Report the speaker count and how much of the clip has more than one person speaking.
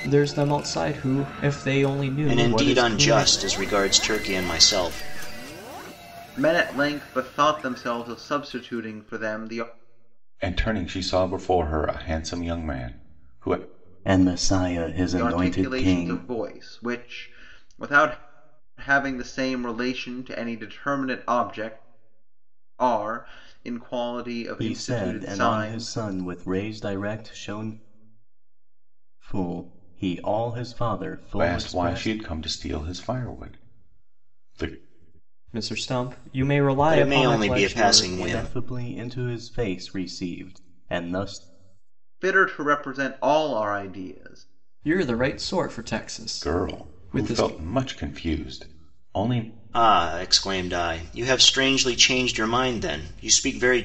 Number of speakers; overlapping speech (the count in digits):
5, about 13%